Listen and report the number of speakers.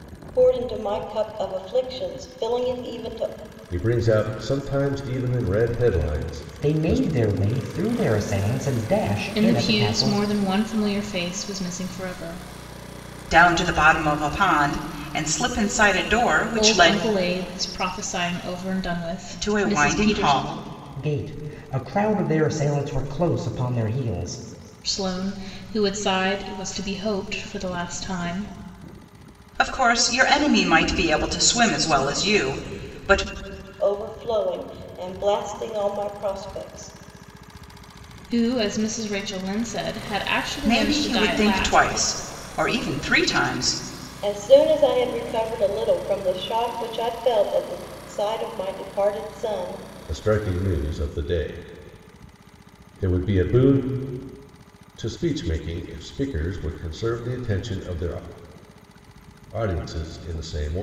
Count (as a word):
five